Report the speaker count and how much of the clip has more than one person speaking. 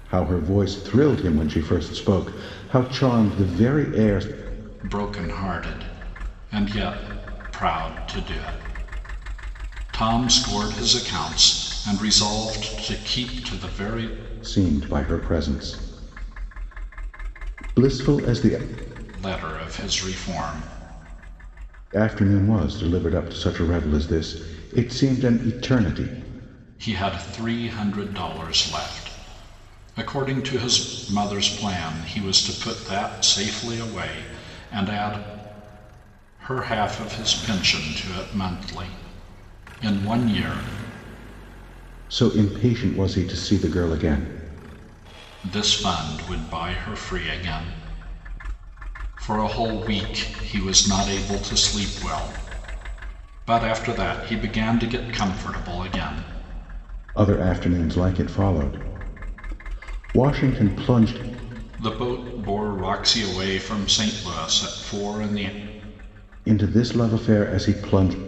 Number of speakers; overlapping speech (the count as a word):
two, no overlap